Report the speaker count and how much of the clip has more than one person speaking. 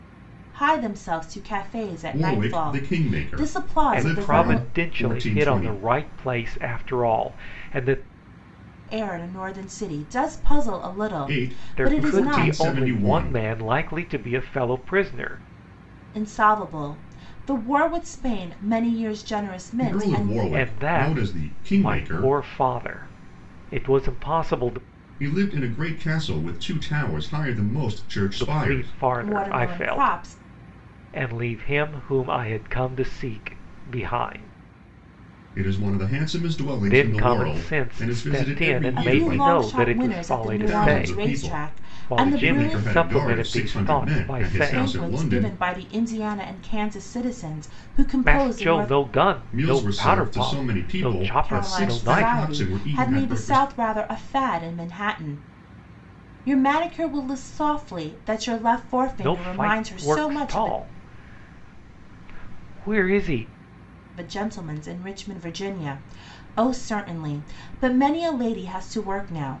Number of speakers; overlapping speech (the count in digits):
3, about 36%